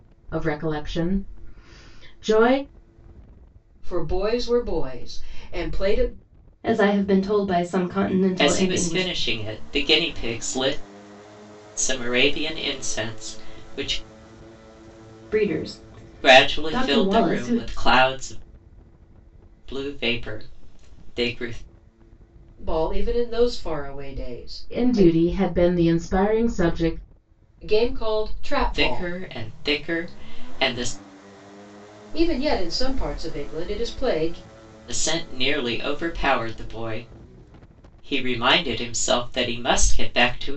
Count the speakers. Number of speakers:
four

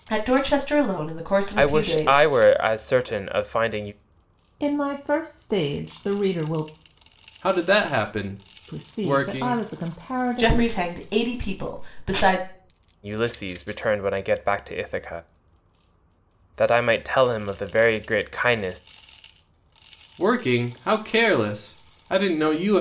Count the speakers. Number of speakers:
four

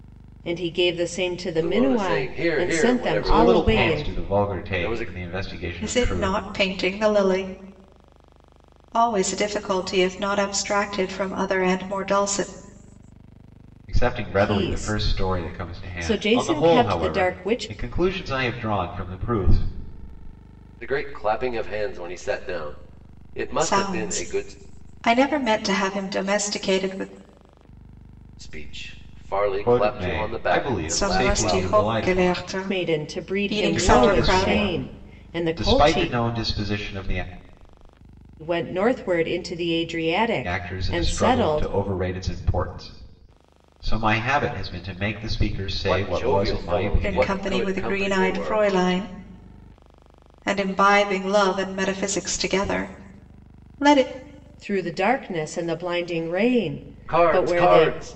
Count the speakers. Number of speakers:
four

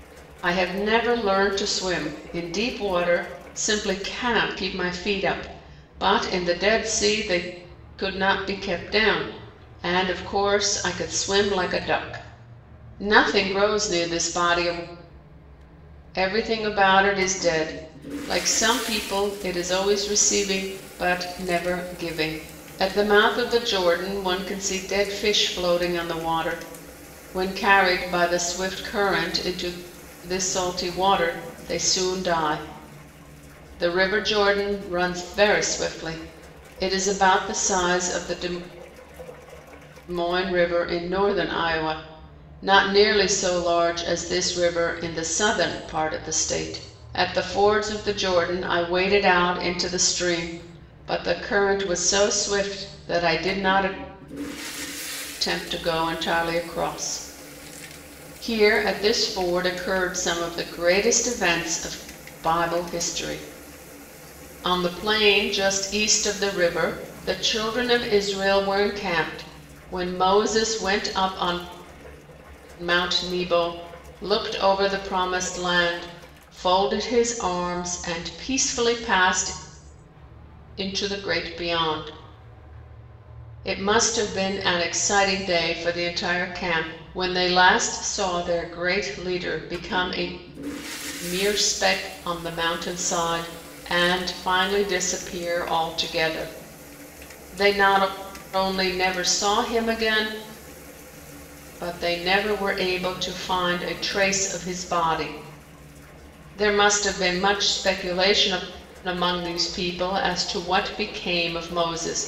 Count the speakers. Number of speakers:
one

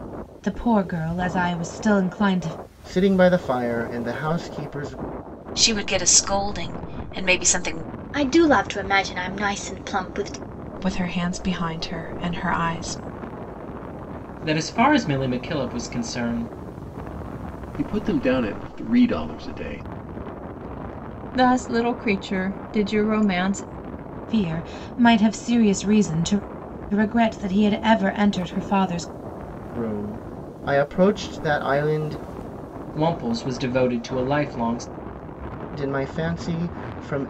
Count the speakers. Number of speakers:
eight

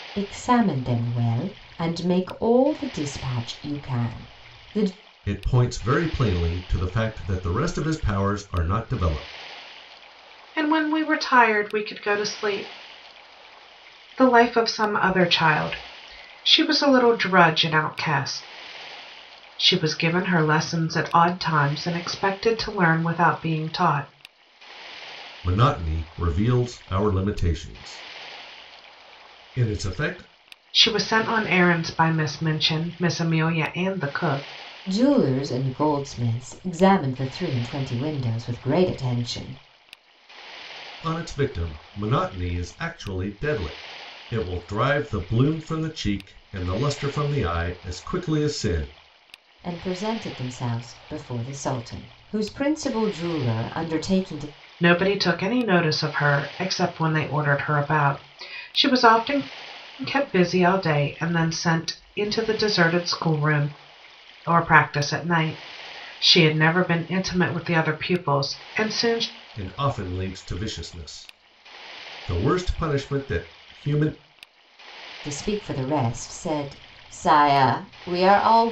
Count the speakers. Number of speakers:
three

